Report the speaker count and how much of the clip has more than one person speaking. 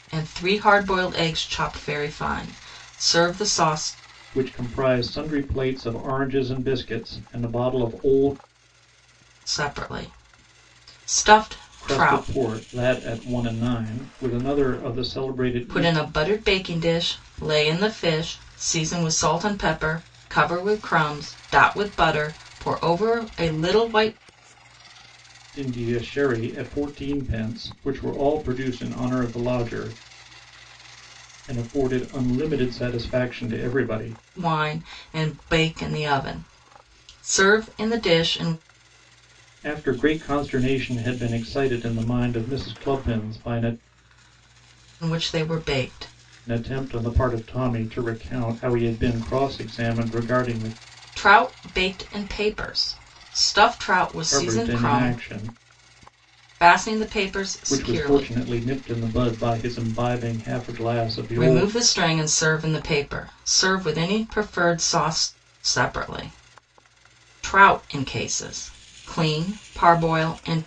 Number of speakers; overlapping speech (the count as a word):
two, about 4%